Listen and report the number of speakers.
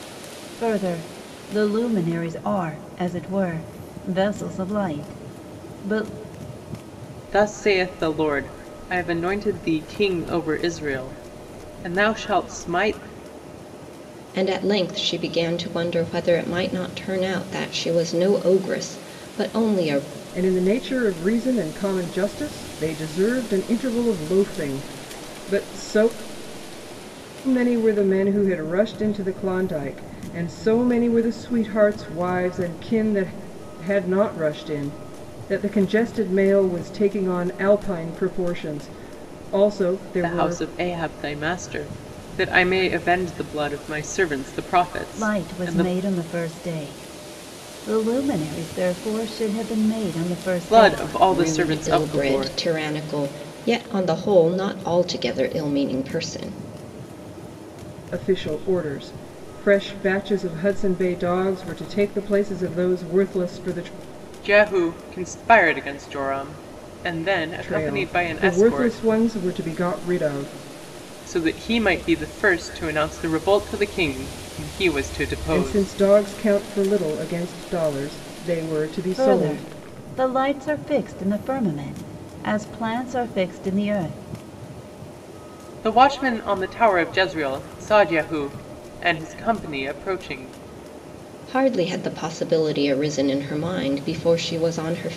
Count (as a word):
four